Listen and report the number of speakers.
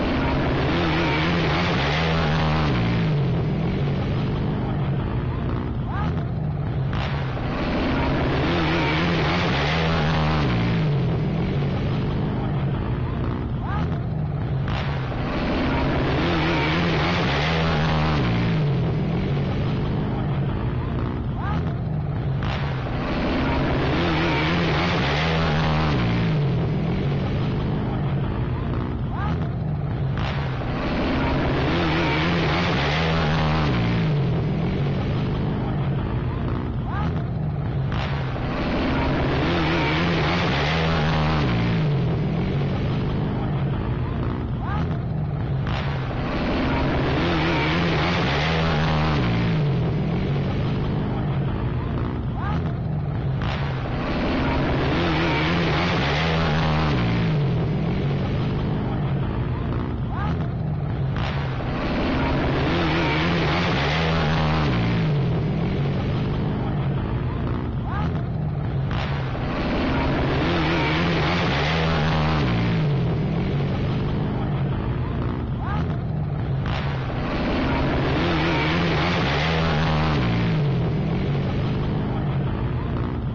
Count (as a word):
zero